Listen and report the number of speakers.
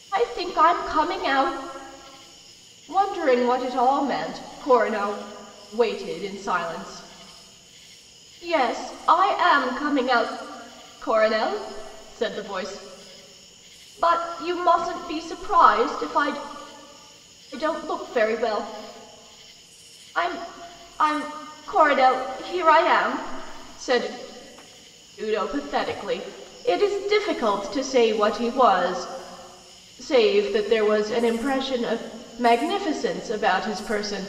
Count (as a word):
one